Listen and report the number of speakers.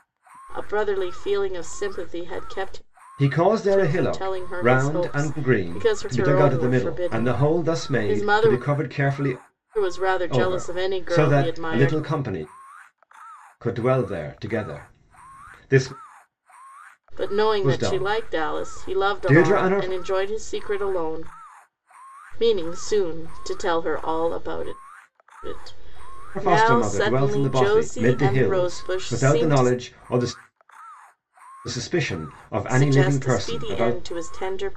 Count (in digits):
2